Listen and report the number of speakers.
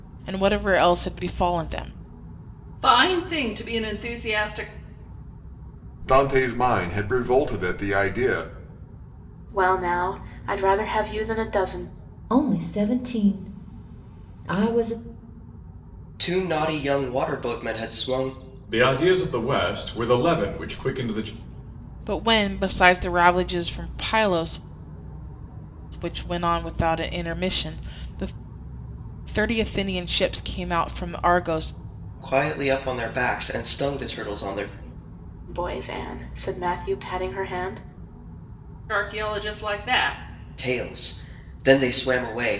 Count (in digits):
7